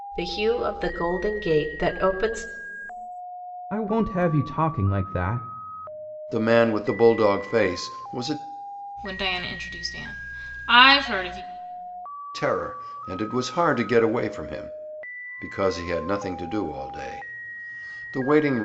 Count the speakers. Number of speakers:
4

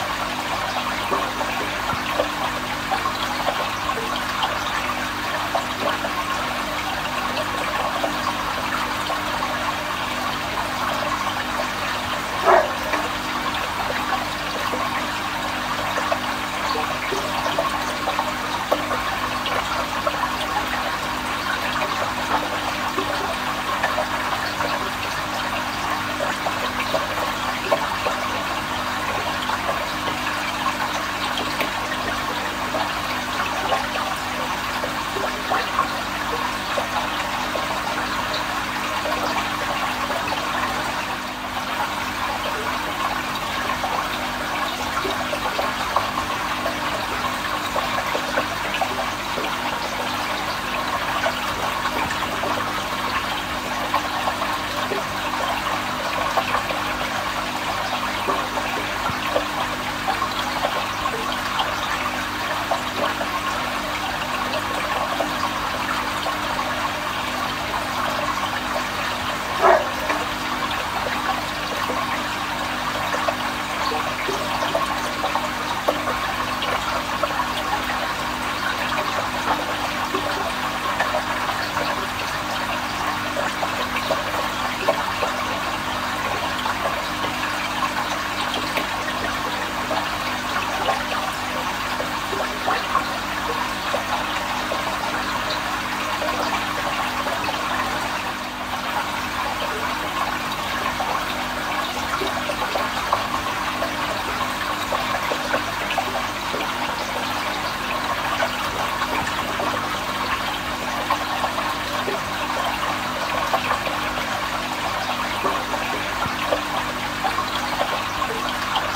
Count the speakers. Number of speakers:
0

